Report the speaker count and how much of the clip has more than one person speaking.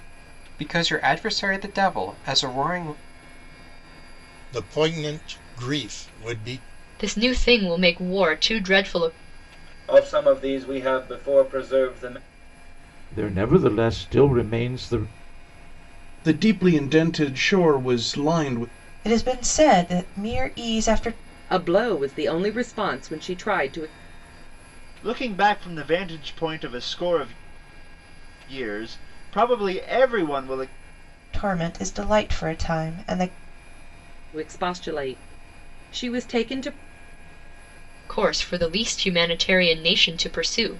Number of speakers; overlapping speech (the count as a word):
nine, no overlap